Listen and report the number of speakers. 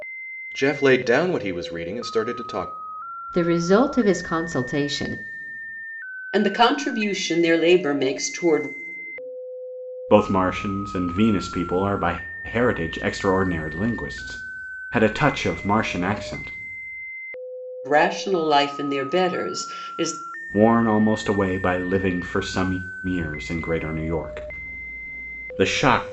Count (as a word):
four